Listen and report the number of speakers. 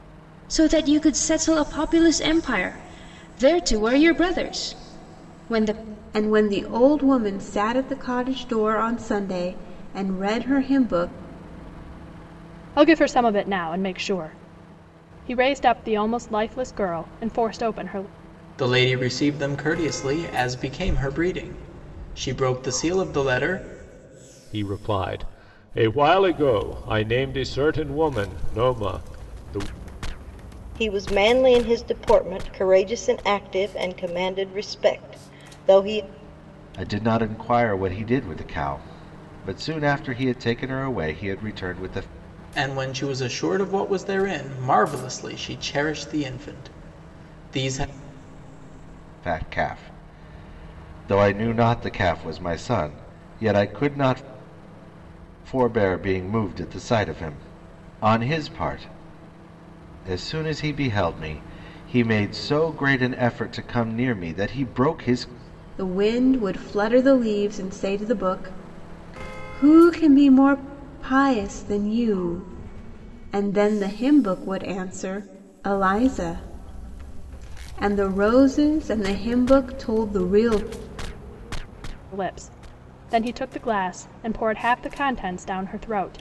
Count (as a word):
seven